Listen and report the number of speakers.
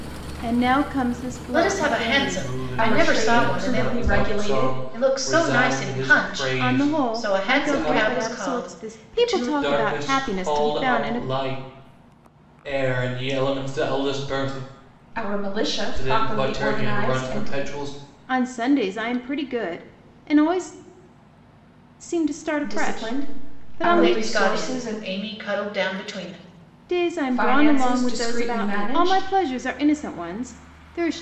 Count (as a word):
four